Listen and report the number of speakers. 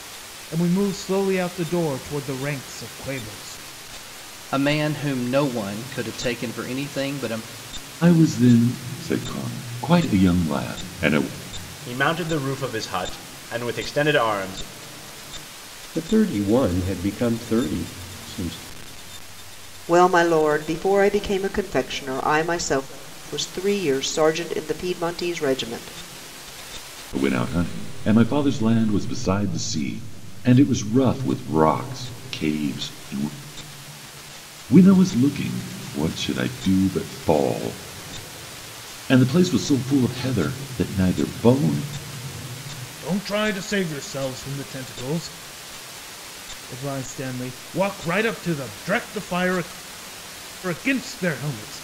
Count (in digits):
6